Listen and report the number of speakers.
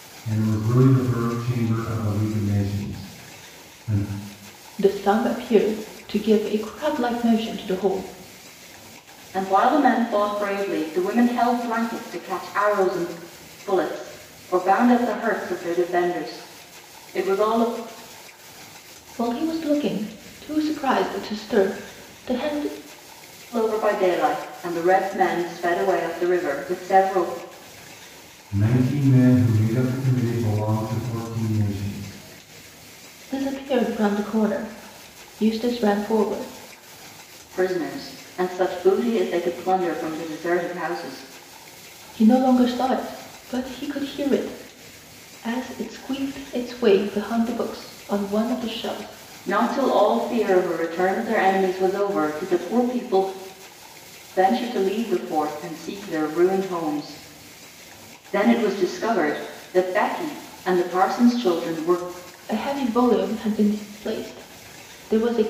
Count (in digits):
3